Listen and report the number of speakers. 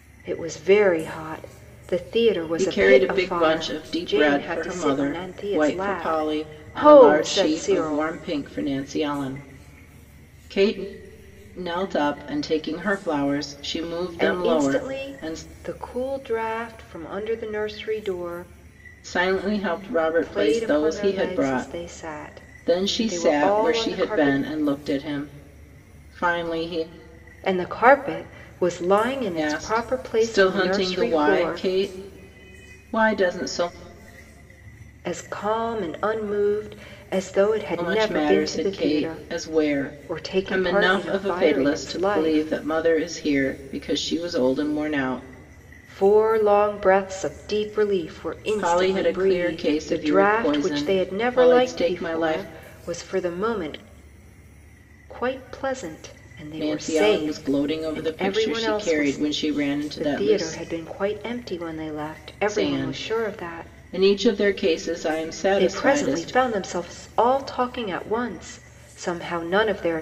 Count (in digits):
2